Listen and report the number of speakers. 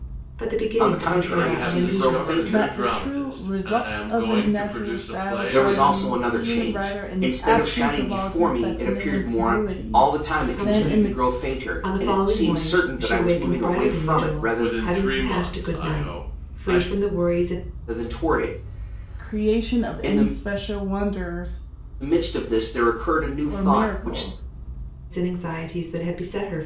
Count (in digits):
4